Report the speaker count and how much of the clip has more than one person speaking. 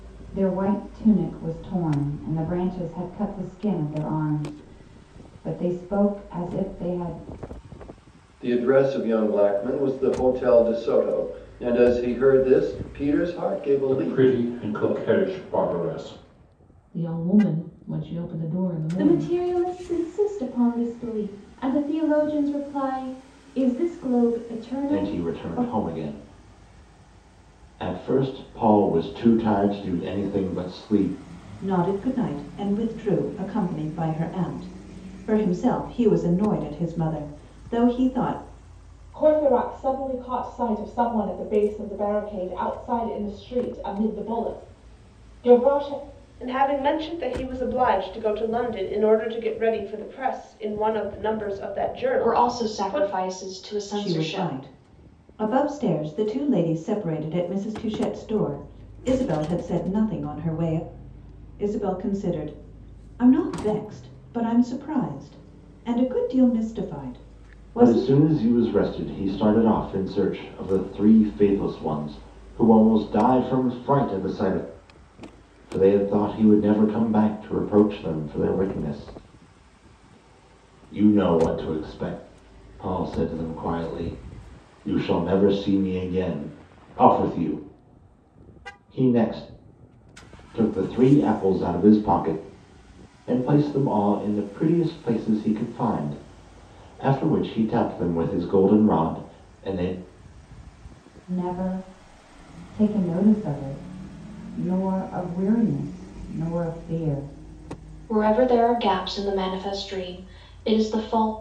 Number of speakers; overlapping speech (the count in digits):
10, about 4%